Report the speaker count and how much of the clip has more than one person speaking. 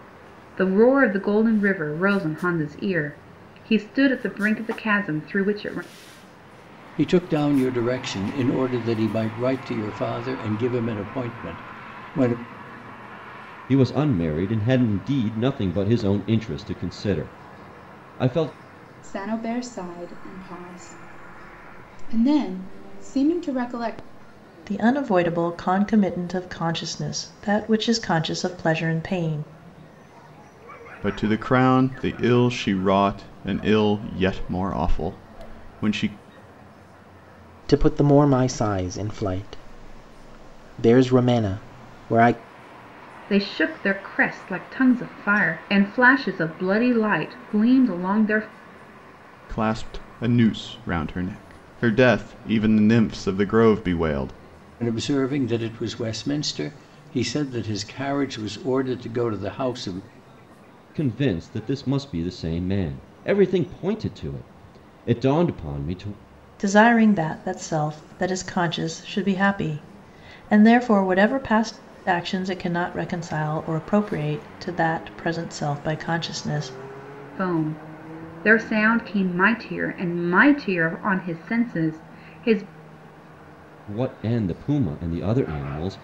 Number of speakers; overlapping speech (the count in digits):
7, no overlap